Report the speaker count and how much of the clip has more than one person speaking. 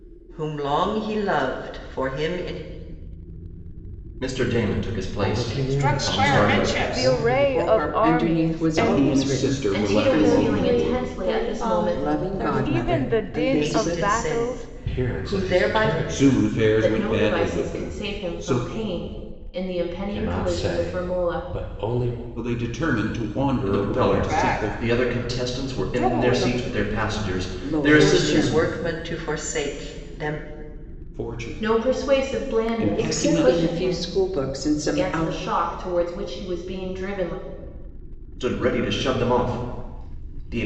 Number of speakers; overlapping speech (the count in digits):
9, about 54%